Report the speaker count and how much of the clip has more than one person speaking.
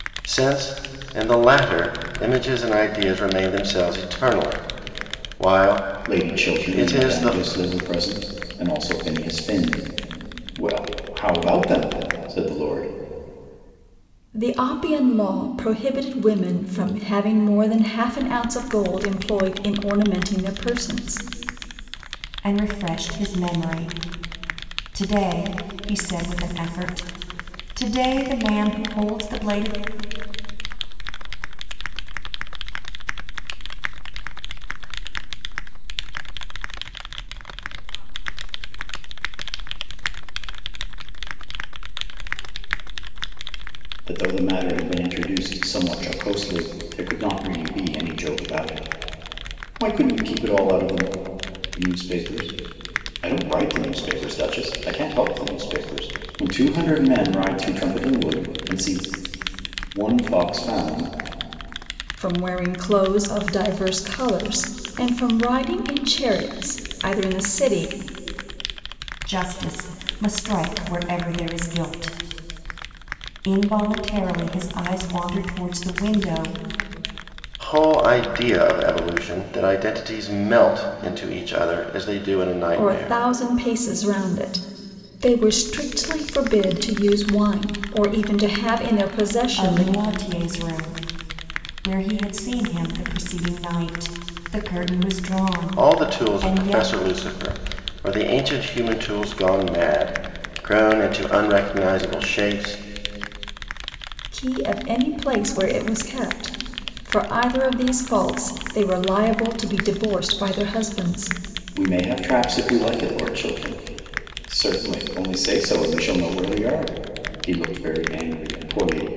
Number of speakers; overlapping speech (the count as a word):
five, about 4%